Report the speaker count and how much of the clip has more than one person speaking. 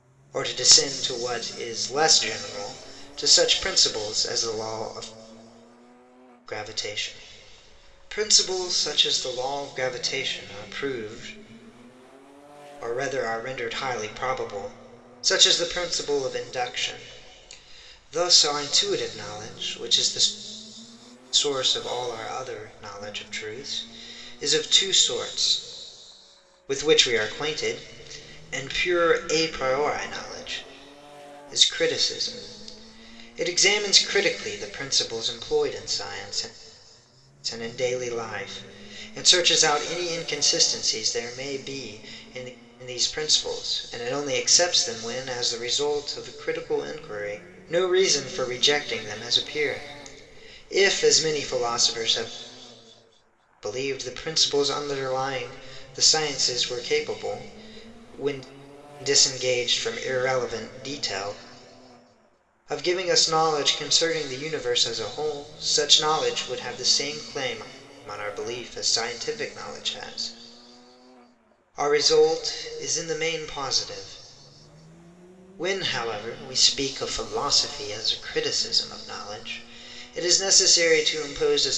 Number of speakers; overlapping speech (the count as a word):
one, no overlap